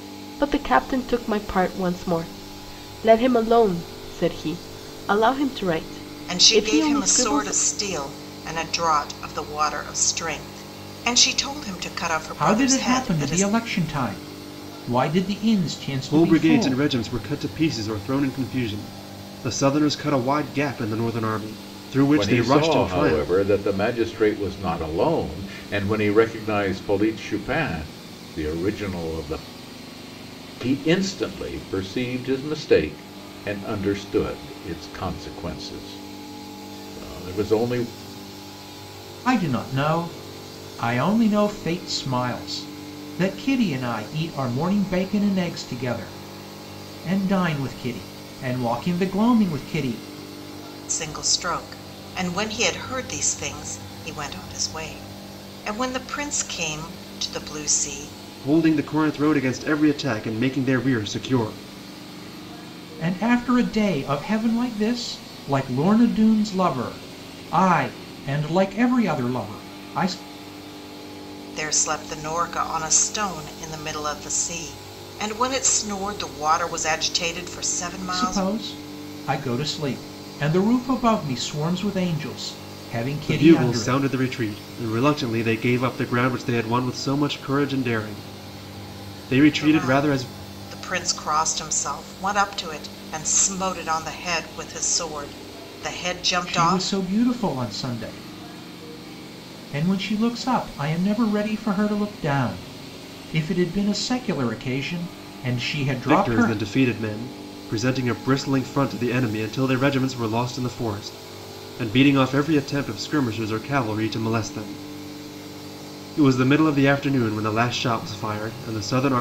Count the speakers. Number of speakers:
5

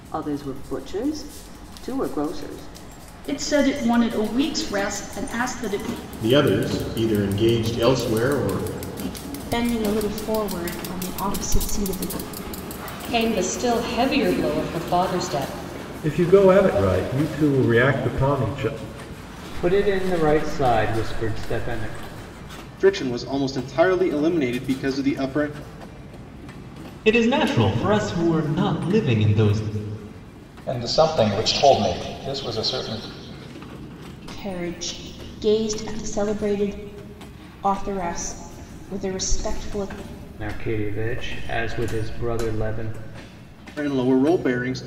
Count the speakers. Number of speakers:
10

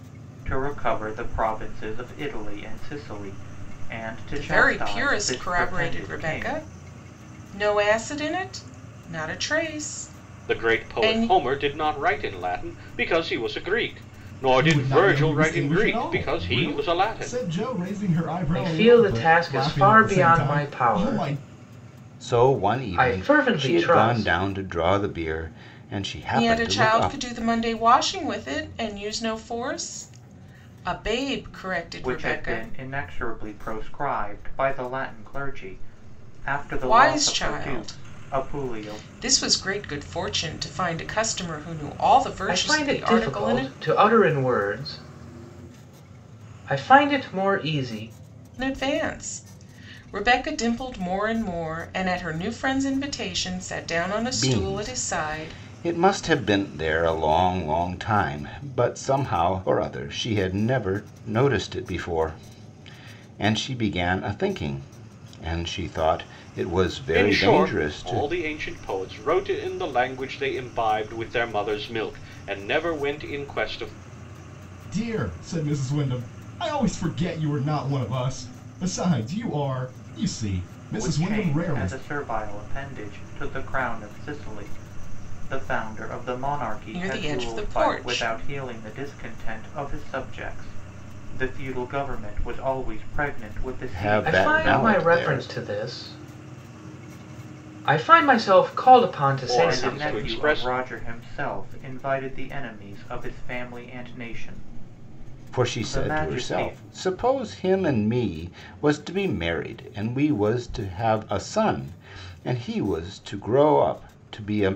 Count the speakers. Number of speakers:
6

